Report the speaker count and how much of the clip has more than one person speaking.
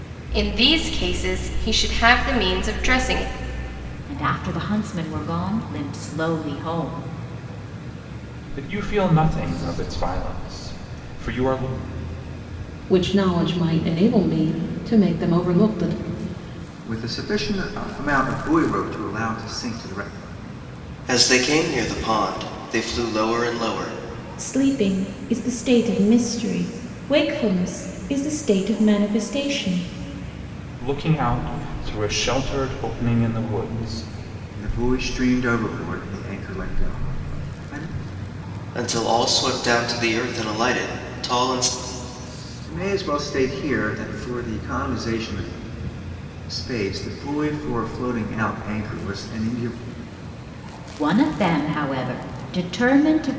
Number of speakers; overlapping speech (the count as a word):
seven, no overlap